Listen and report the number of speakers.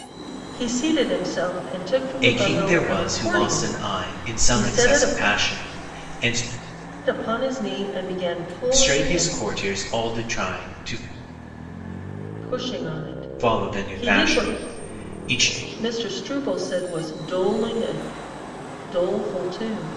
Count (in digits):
2